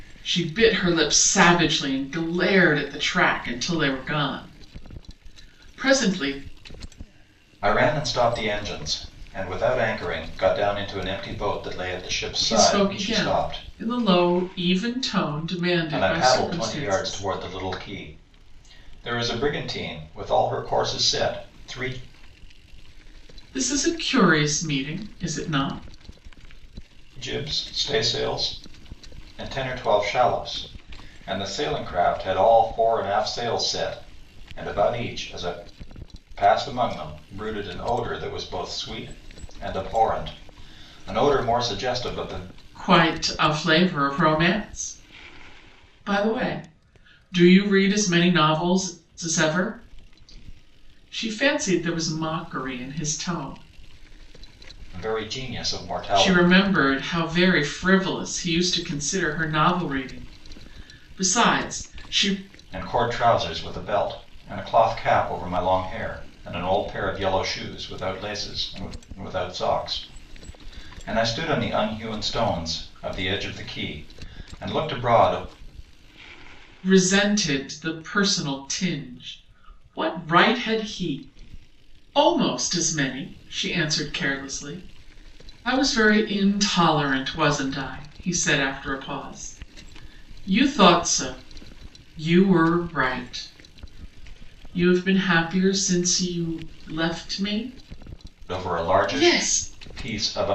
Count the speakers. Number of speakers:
two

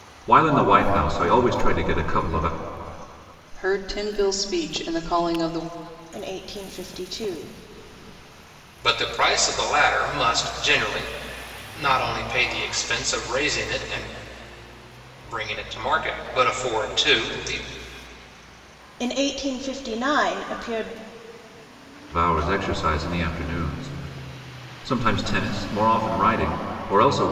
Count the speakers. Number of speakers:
four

